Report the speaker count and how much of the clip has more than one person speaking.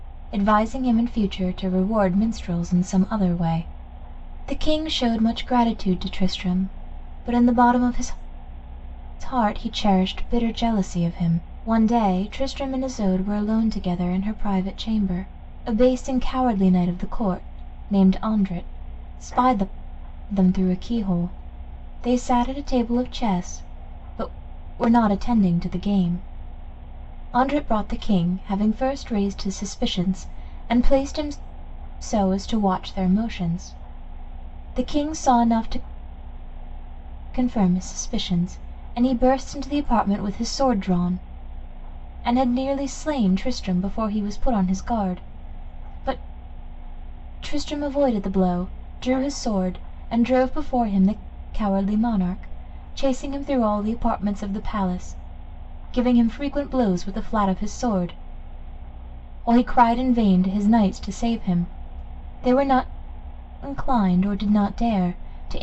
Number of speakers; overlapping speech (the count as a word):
one, no overlap